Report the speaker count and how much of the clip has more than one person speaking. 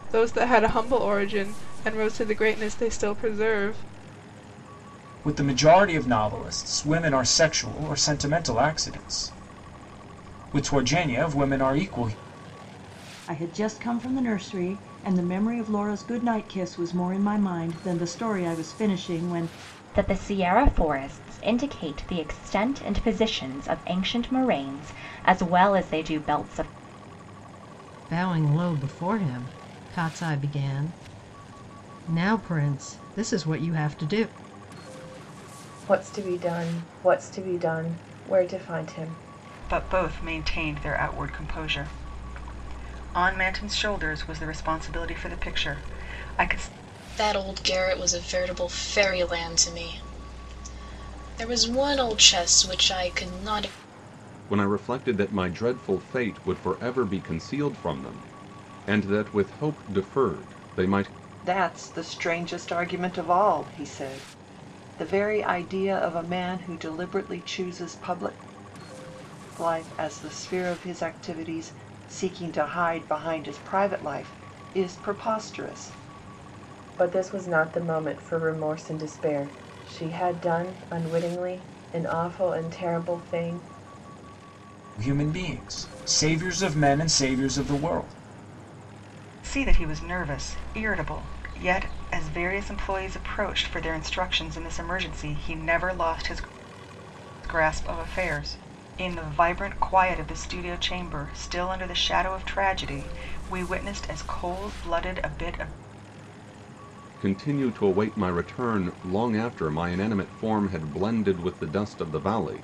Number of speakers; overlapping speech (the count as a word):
ten, no overlap